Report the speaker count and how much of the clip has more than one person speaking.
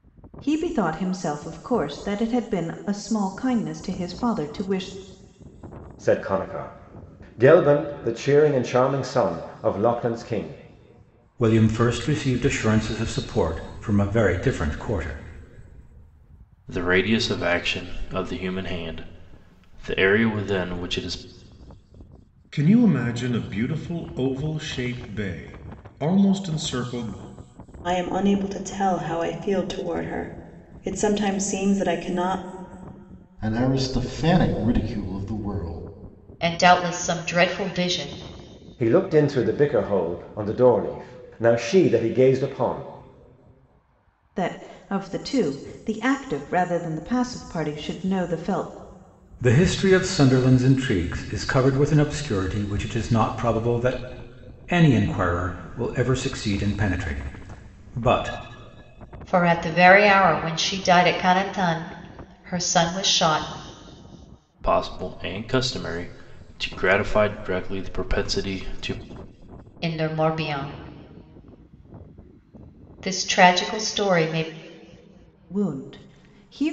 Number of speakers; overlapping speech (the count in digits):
8, no overlap